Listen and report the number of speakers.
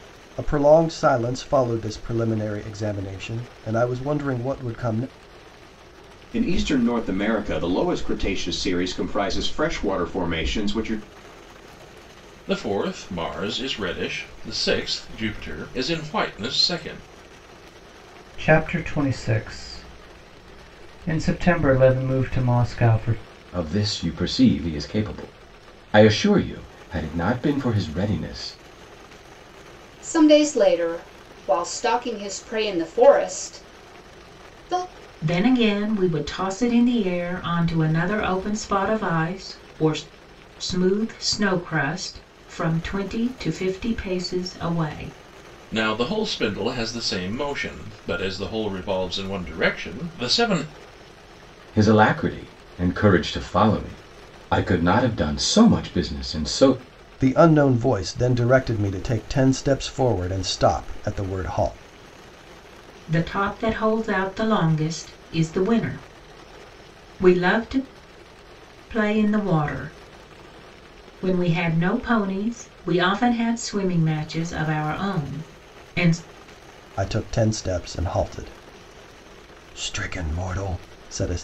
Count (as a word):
seven